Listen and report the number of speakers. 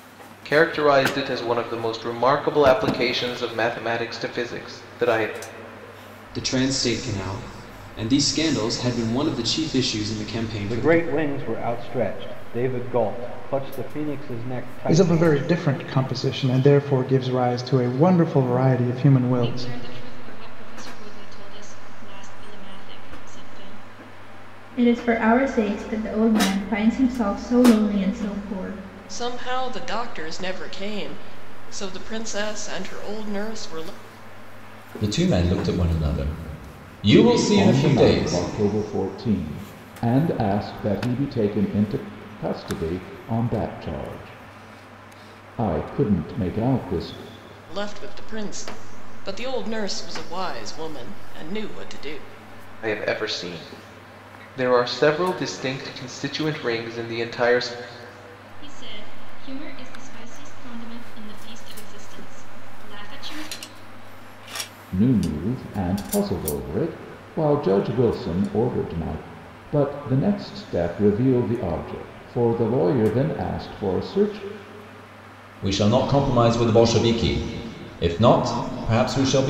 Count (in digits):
9